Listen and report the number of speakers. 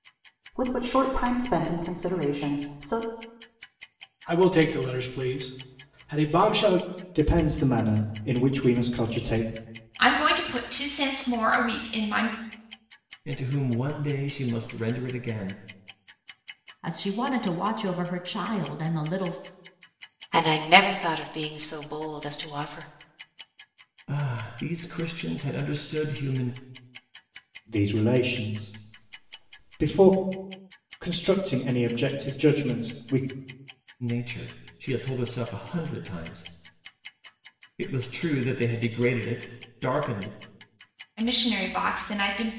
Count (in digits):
7